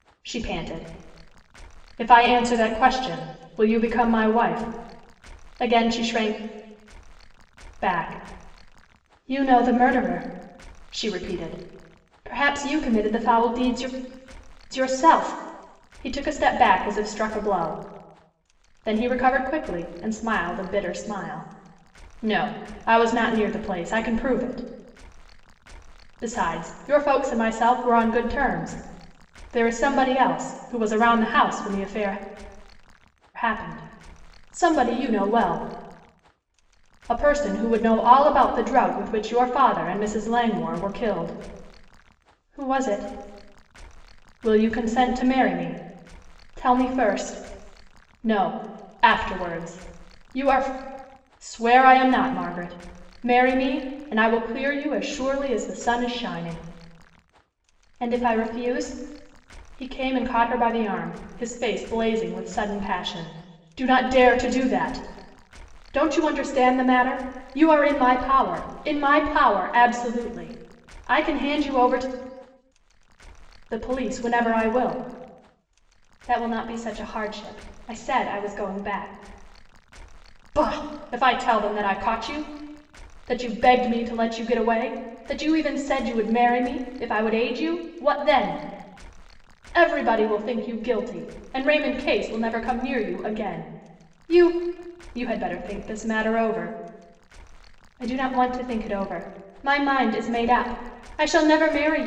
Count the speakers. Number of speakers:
one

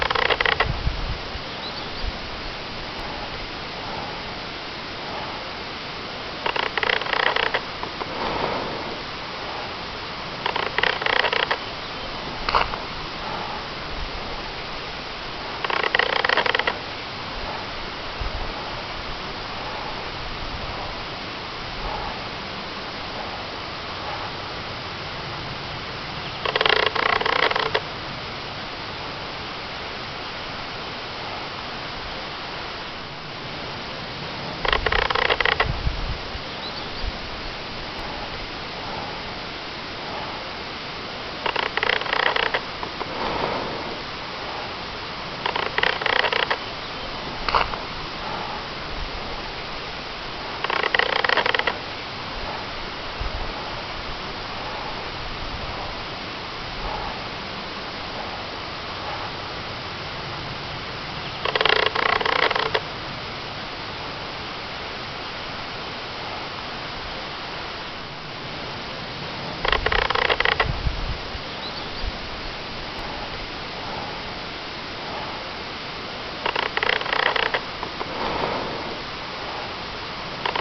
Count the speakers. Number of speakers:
zero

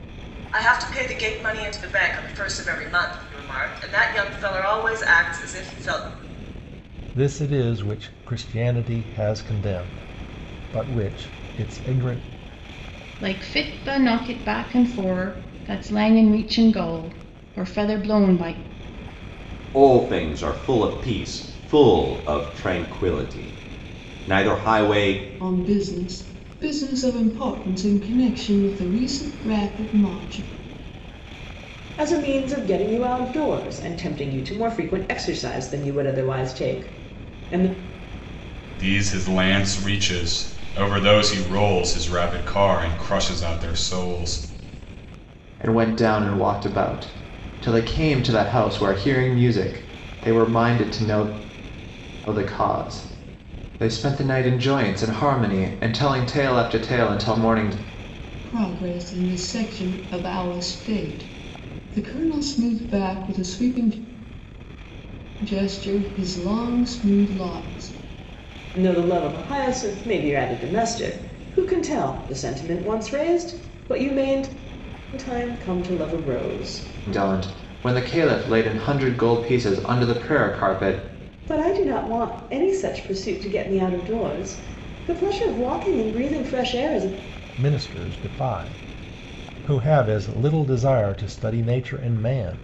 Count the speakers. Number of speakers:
eight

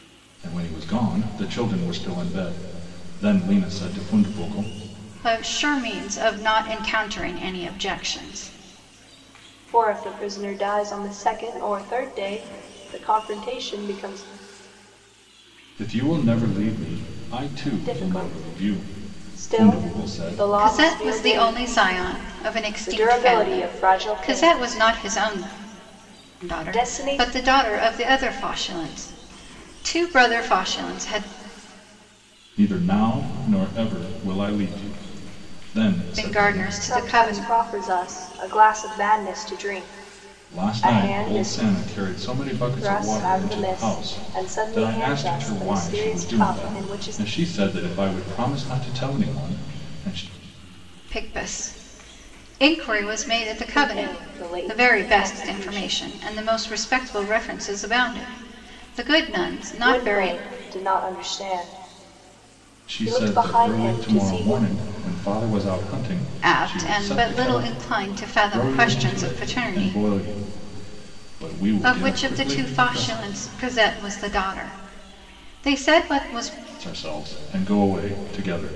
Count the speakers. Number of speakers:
three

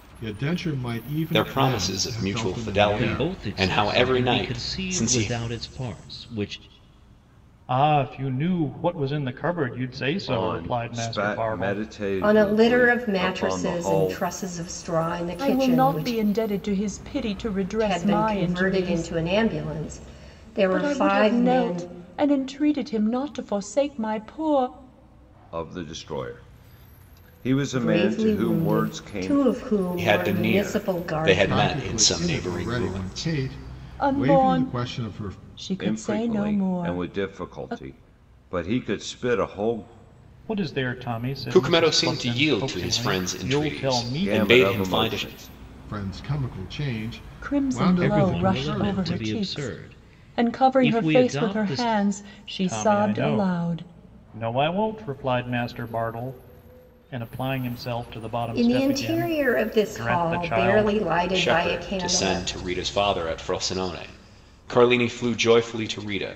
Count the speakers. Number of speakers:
seven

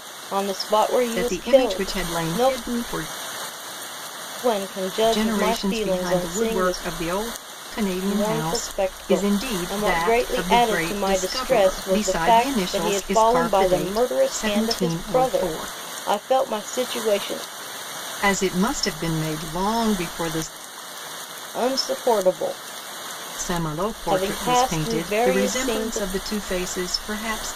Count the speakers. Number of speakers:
two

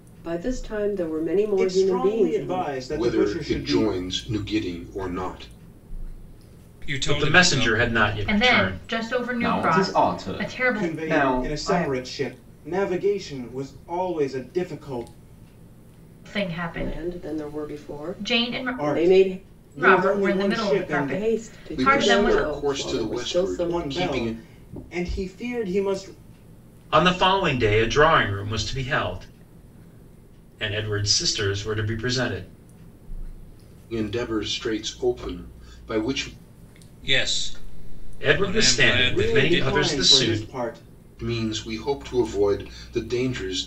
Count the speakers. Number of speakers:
seven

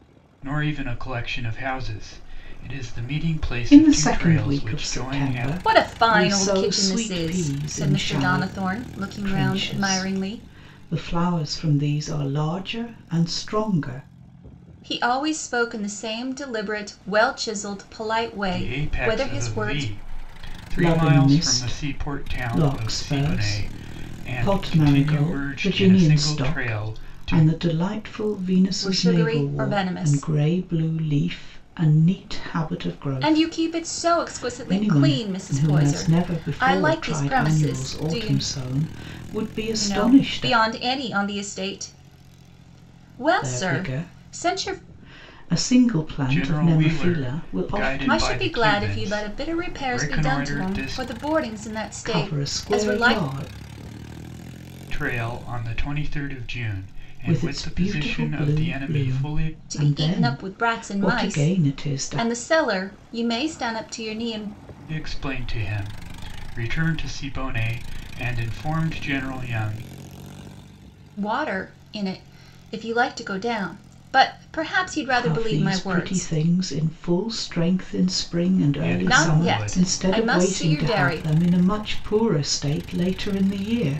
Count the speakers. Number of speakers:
three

